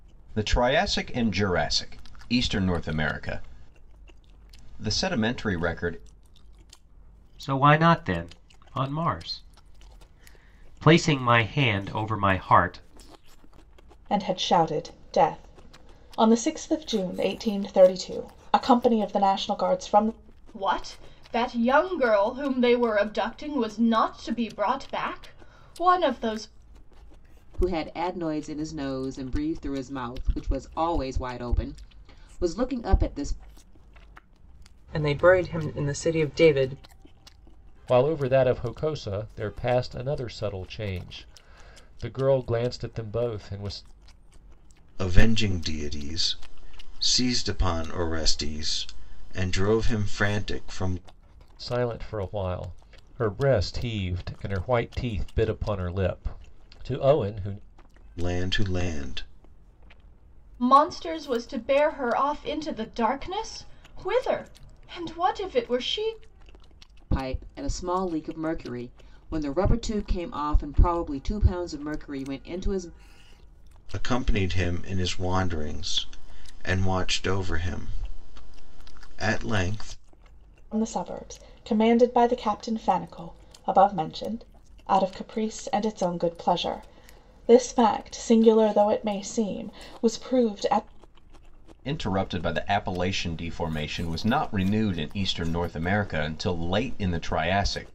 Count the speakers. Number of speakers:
eight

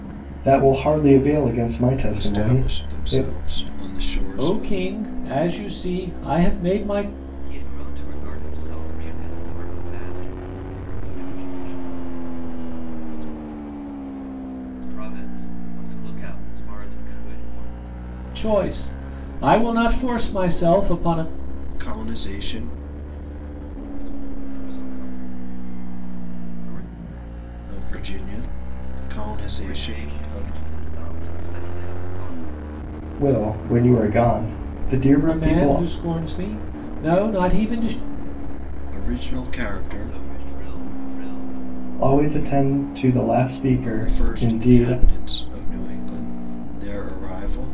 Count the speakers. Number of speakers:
four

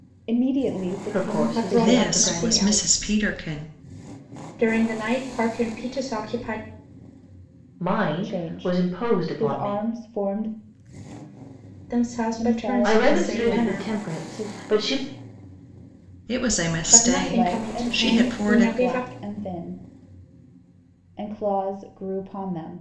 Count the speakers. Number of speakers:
four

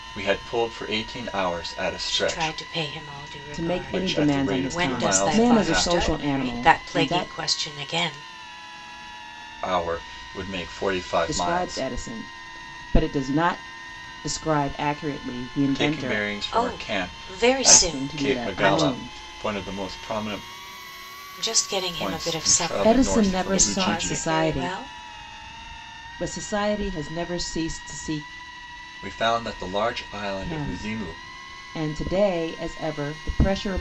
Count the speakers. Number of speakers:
three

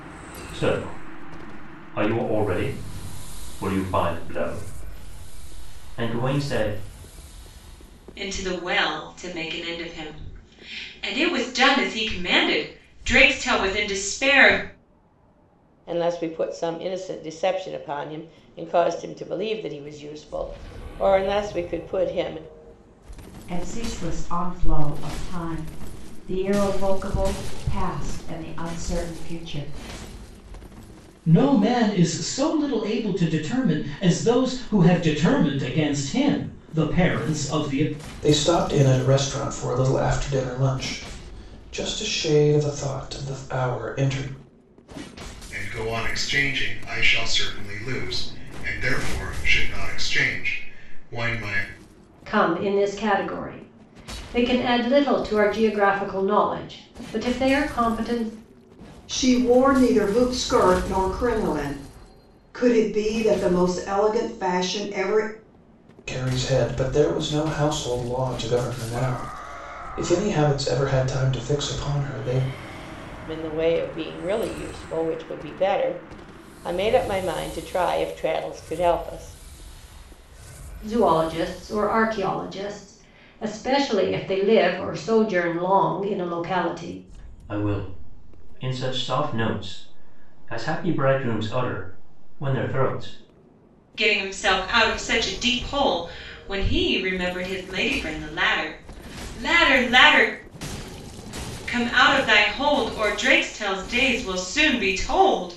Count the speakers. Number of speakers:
nine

